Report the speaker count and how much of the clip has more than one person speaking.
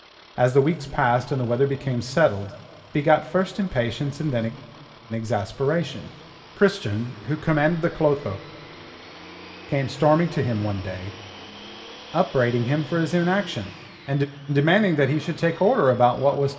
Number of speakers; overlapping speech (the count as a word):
one, no overlap